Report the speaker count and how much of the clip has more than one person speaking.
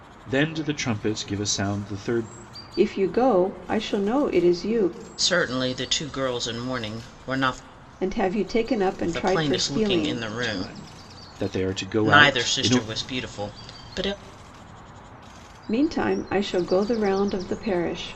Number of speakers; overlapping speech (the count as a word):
three, about 13%